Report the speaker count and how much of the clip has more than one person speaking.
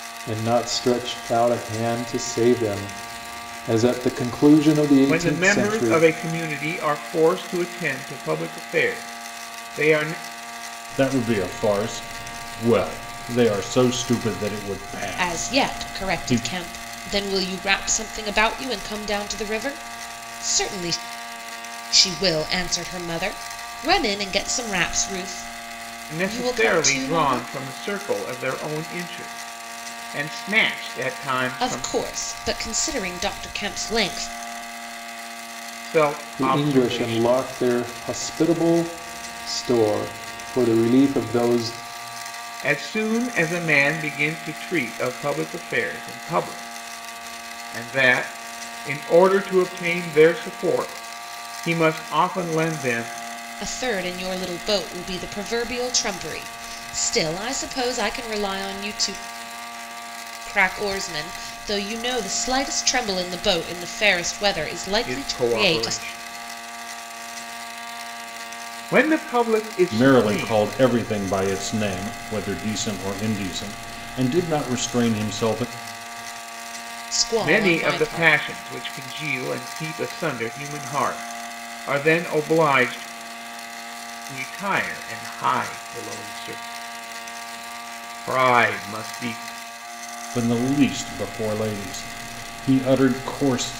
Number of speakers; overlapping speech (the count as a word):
four, about 8%